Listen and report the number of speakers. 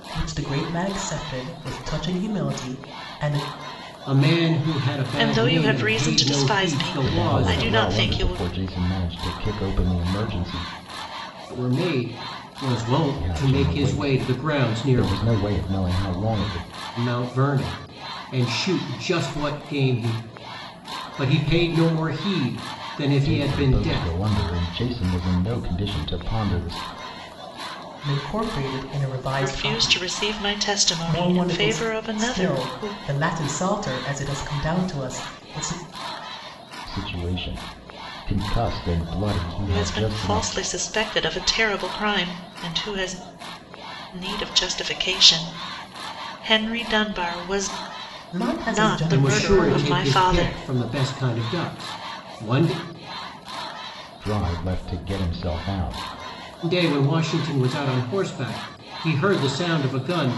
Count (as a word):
four